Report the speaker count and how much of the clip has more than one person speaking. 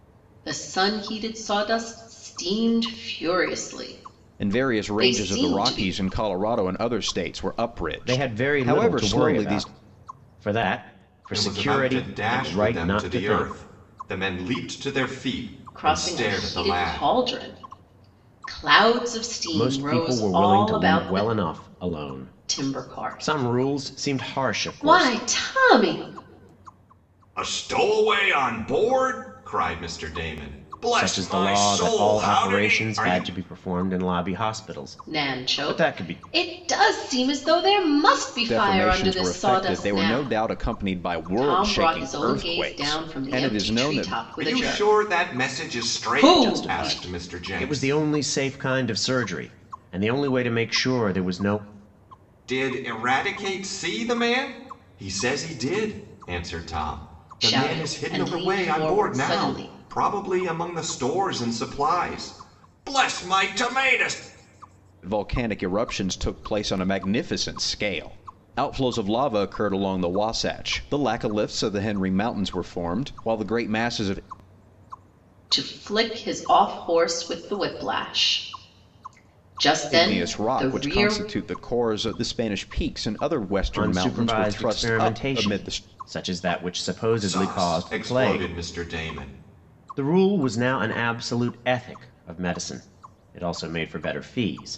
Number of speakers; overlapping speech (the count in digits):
4, about 32%